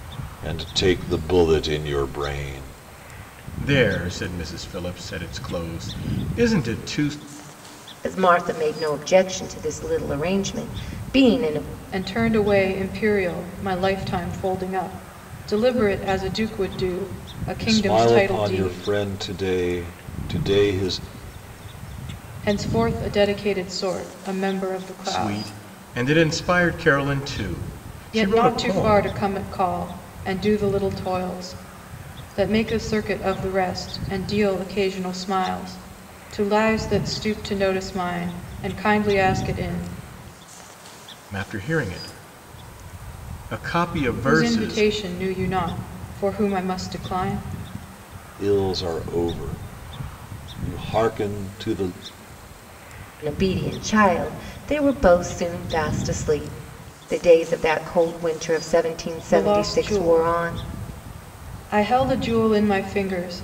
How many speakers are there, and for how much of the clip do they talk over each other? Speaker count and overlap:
four, about 8%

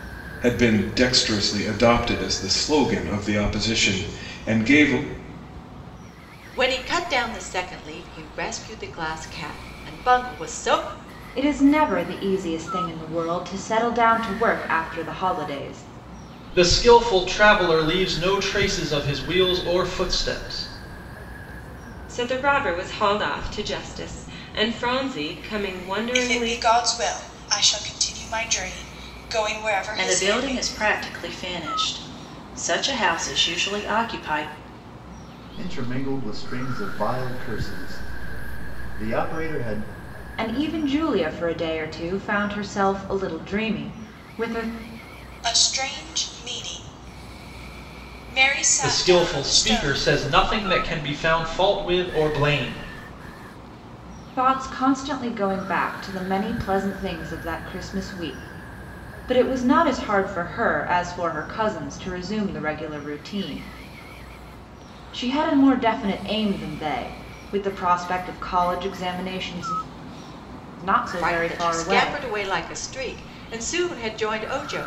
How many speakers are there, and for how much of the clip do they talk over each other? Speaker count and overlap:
eight, about 5%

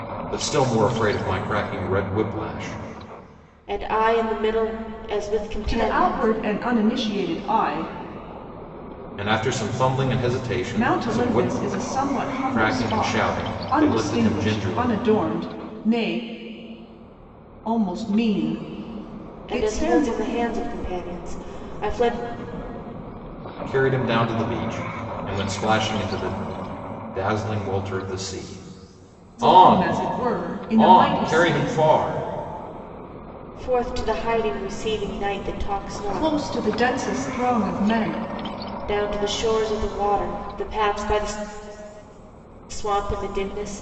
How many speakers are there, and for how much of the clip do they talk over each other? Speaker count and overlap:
three, about 14%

